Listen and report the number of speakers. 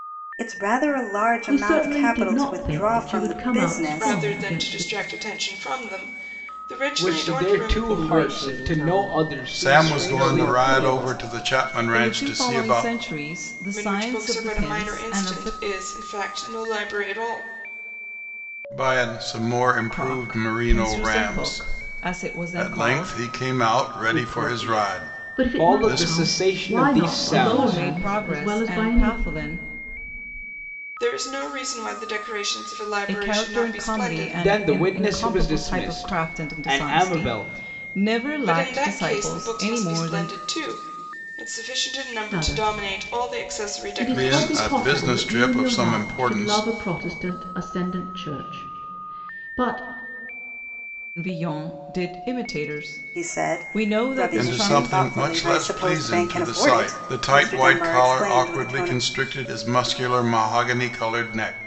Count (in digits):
7